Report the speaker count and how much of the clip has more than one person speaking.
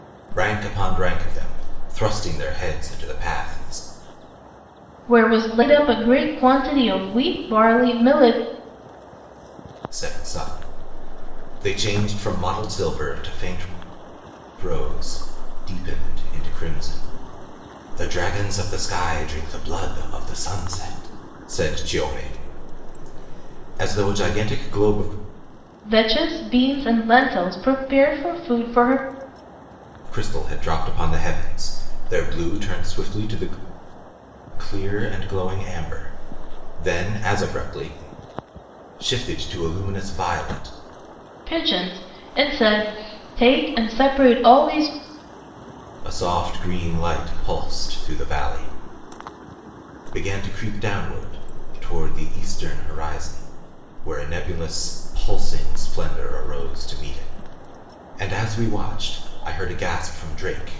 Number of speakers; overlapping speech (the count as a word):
two, no overlap